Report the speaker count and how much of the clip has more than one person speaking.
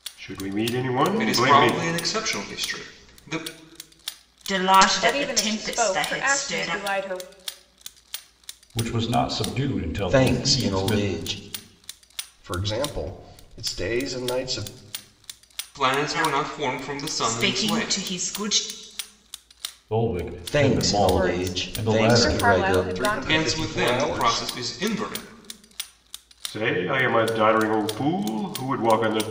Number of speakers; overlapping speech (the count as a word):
seven, about 32%